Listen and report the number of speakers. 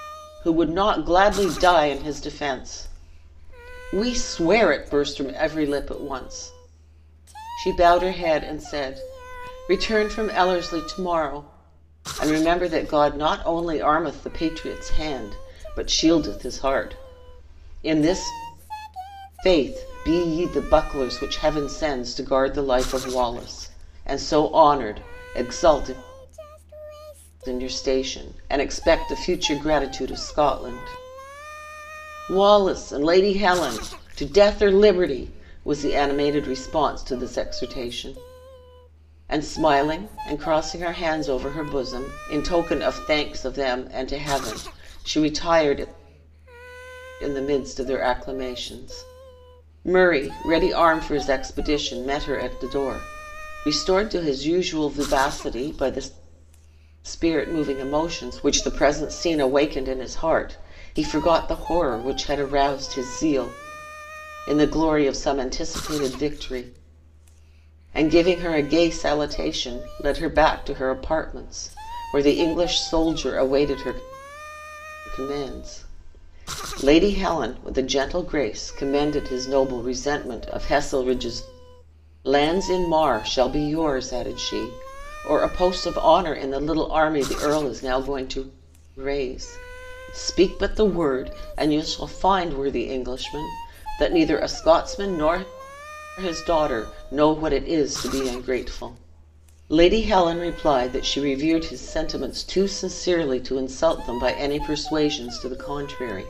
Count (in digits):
1